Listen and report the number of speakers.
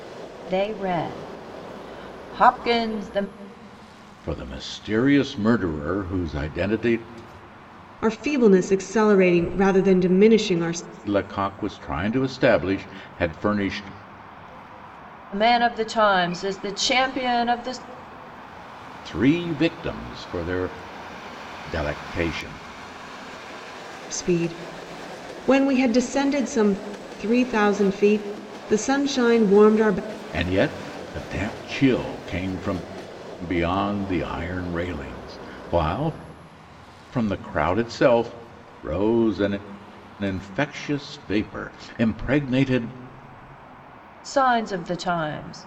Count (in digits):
3